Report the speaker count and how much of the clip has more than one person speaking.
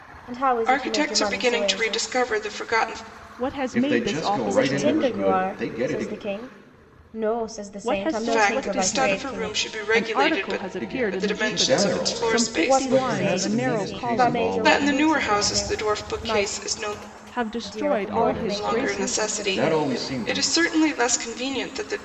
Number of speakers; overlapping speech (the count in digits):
4, about 69%